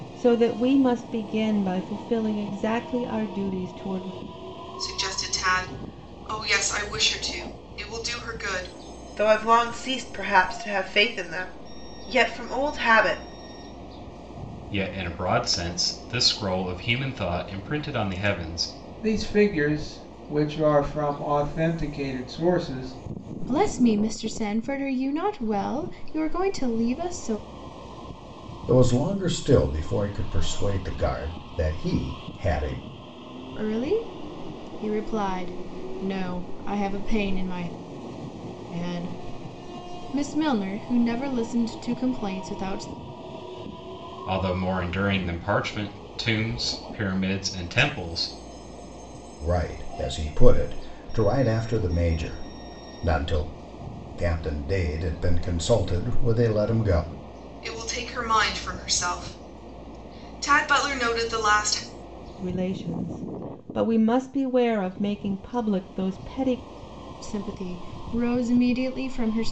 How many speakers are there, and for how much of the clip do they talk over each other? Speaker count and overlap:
seven, no overlap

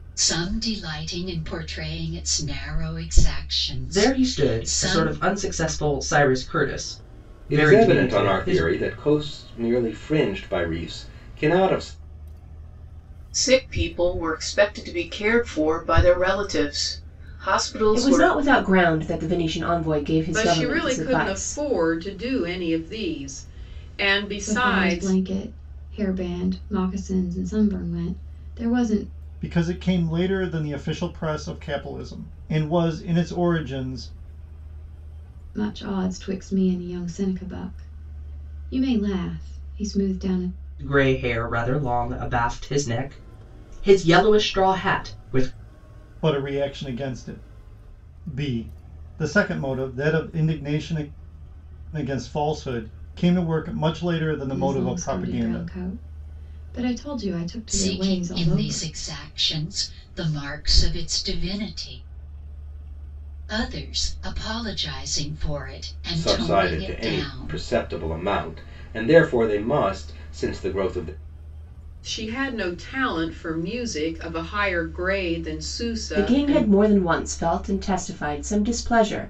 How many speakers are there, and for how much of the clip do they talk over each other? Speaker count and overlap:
eight, about 12%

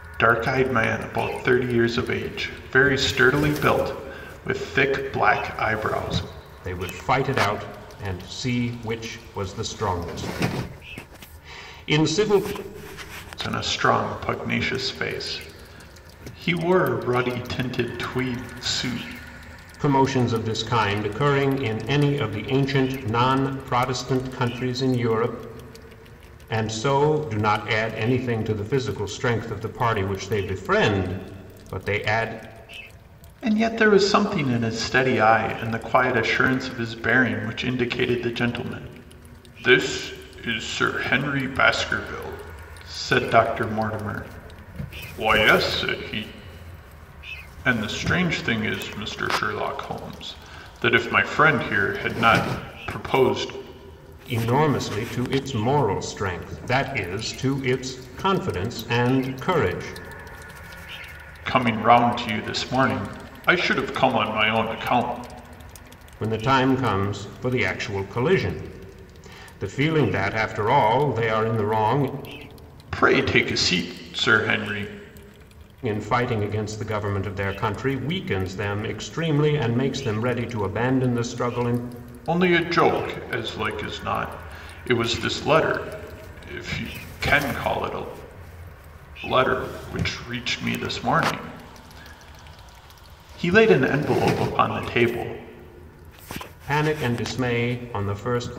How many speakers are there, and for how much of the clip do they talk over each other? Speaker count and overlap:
two, no overlap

